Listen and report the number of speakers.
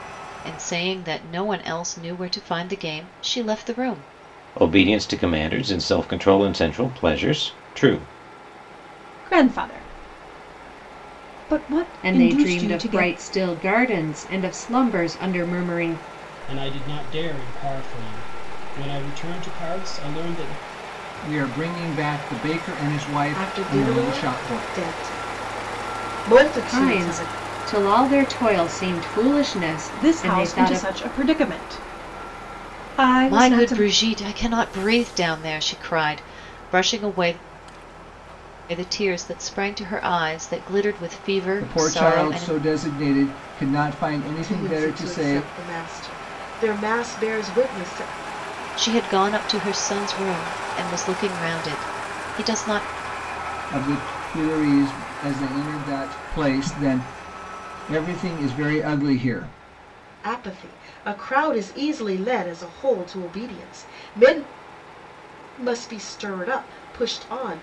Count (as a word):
seven